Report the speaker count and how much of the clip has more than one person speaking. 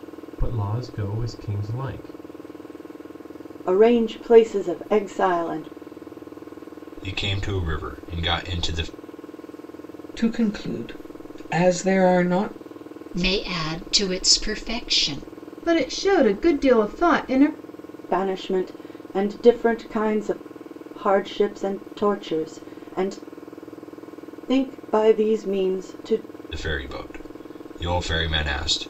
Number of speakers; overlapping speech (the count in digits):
6, no overlap